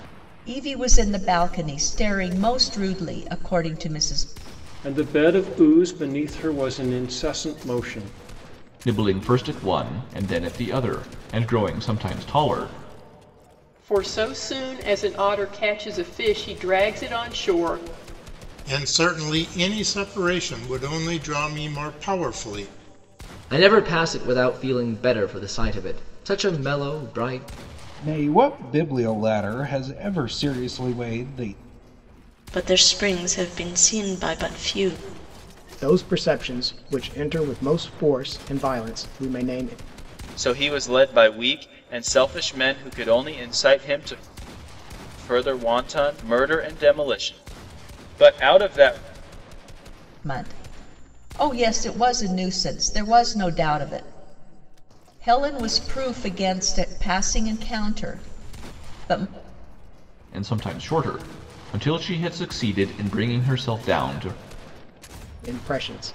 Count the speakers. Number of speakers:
10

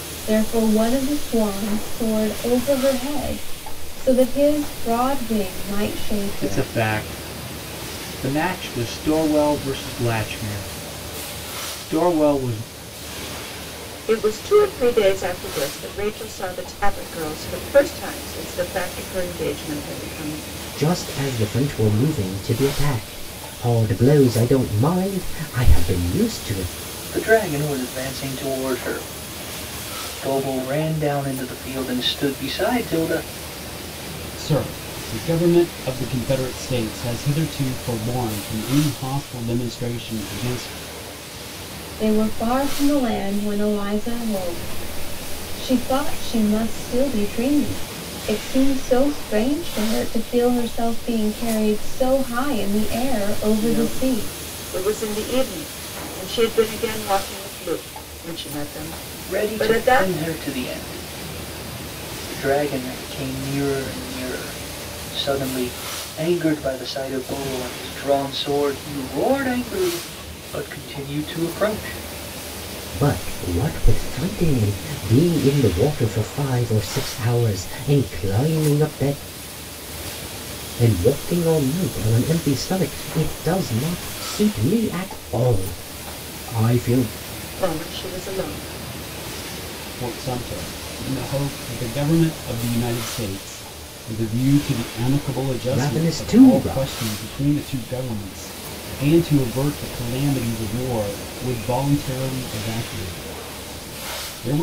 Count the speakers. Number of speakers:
6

